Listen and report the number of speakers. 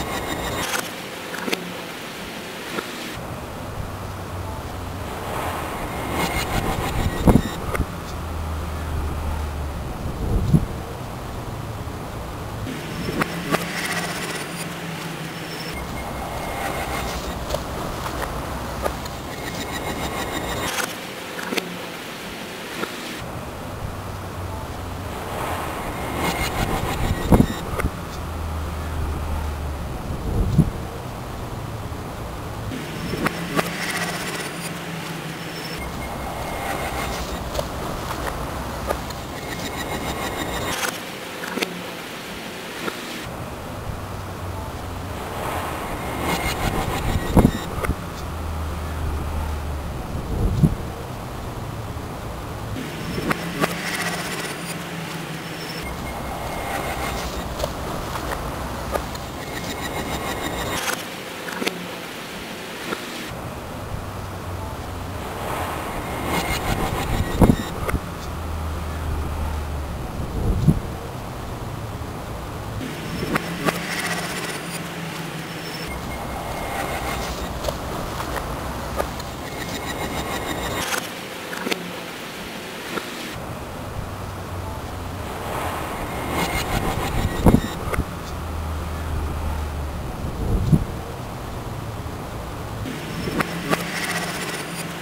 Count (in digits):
0